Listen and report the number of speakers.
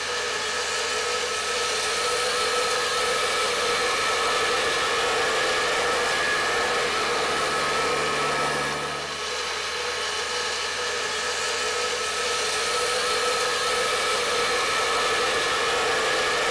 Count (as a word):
zero